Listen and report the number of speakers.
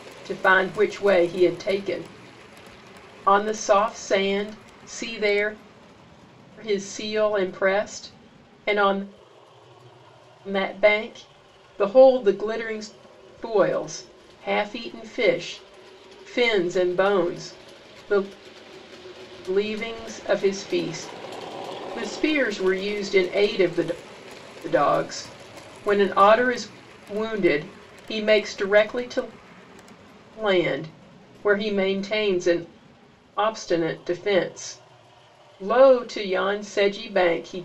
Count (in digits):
1